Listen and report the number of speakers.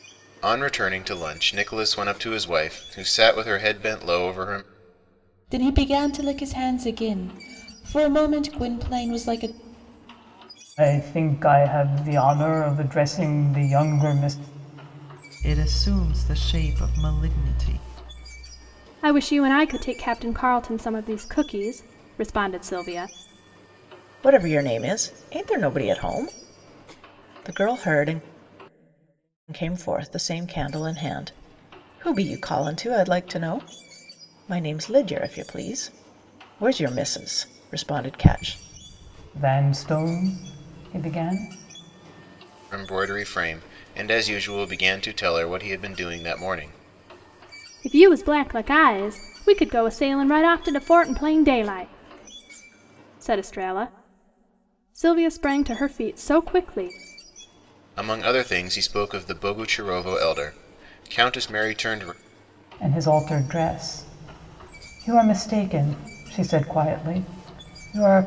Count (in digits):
6